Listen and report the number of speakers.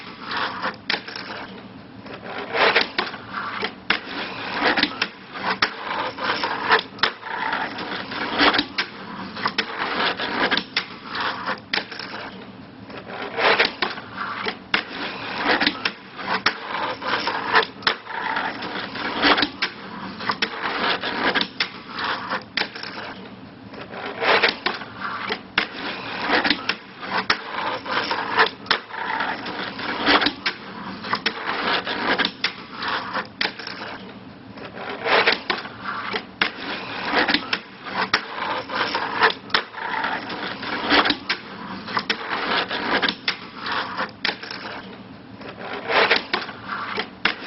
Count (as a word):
zero